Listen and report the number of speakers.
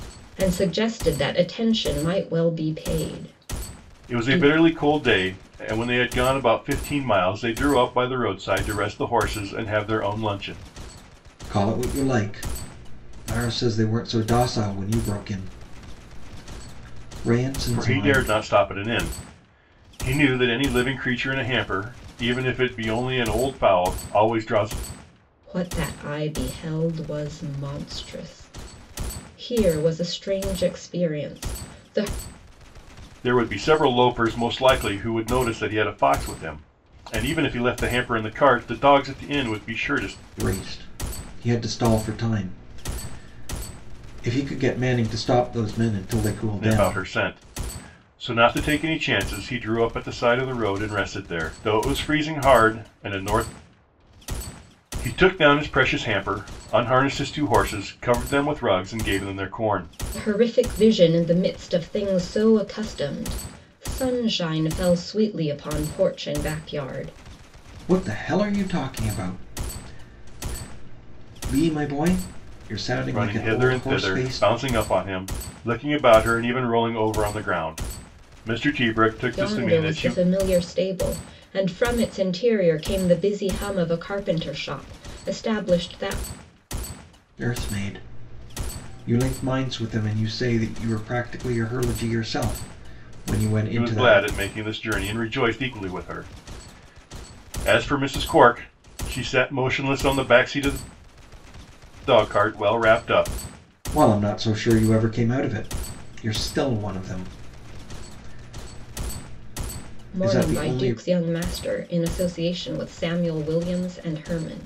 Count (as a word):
three